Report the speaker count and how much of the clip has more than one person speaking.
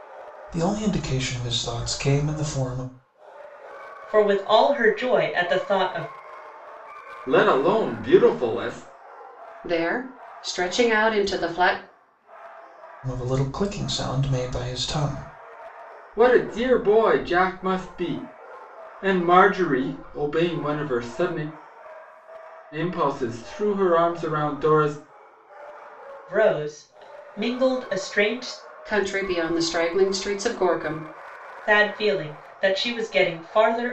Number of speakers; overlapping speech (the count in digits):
4, no overlap